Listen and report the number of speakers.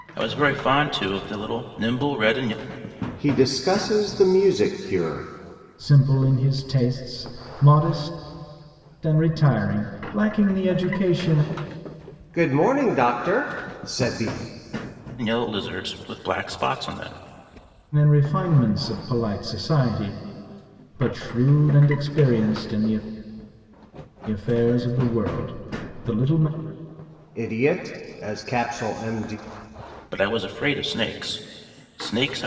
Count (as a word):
three